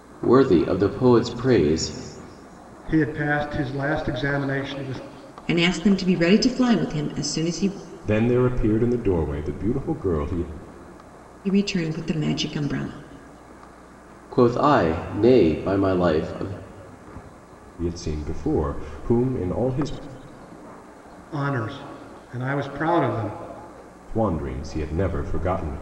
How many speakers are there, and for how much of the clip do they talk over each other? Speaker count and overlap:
4, no overlap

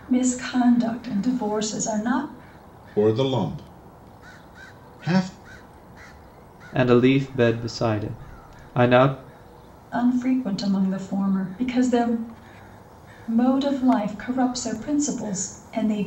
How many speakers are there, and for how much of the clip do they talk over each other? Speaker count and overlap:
3, no overlap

